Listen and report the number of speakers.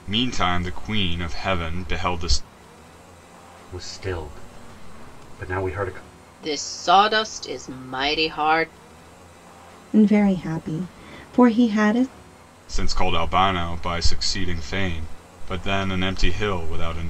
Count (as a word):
four